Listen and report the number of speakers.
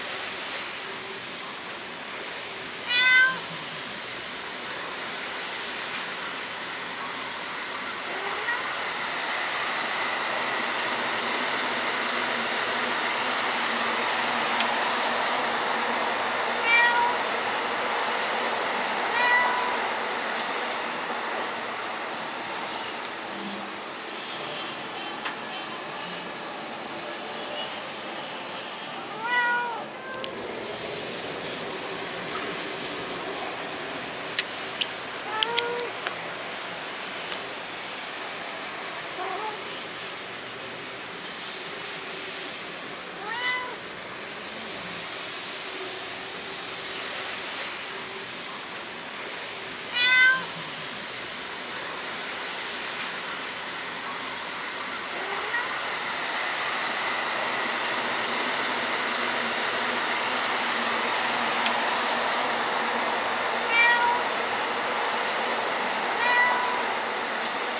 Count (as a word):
zero